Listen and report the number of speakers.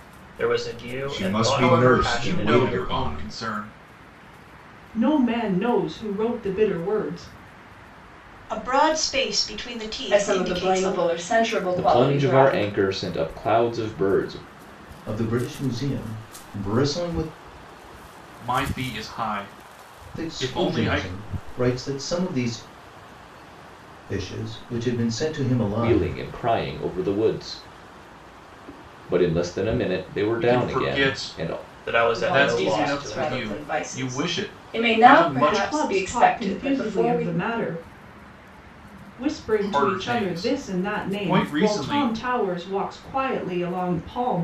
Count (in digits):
8